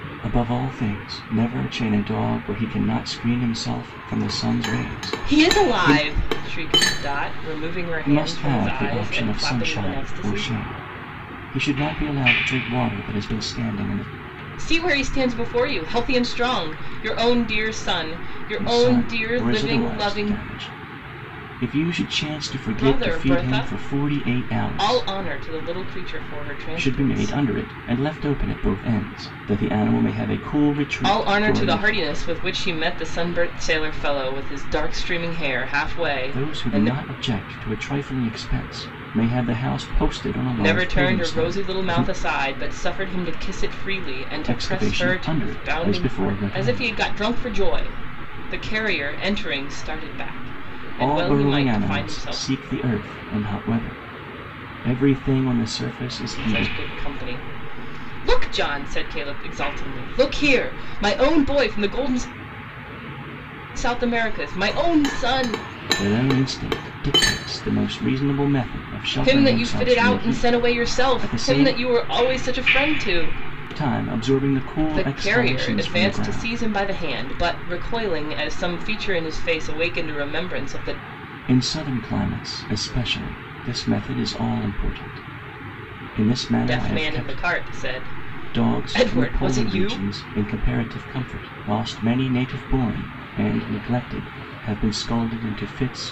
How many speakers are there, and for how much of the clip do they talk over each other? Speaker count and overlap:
2, about 25%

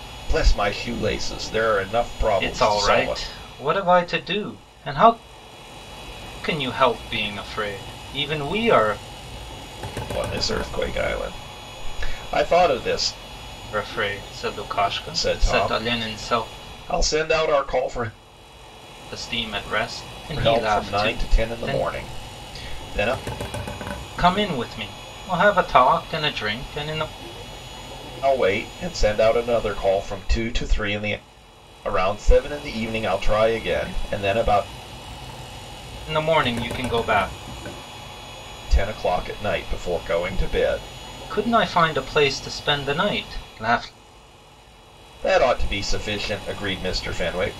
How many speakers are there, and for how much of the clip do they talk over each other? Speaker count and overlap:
2, about 8%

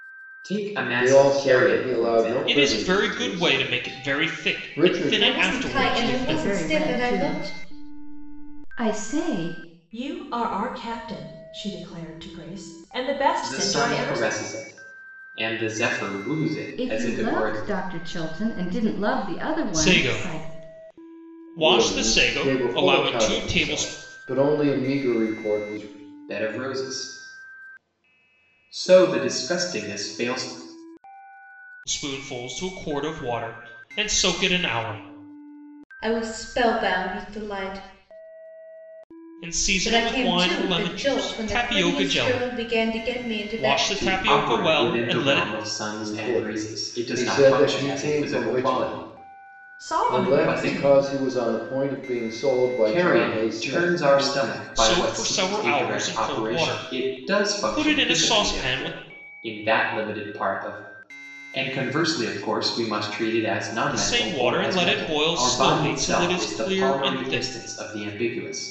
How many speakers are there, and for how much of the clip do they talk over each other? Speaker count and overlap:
6, about 45%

